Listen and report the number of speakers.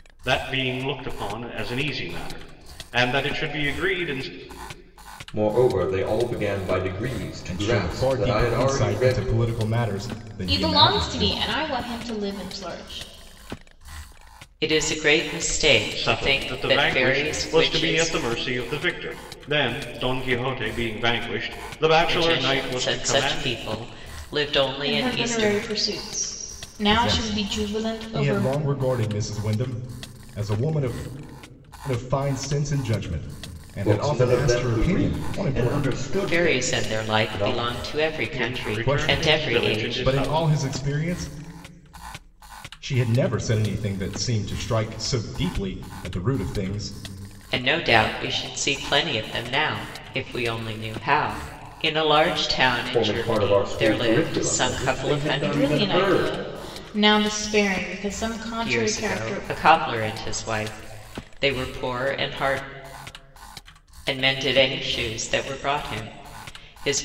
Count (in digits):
5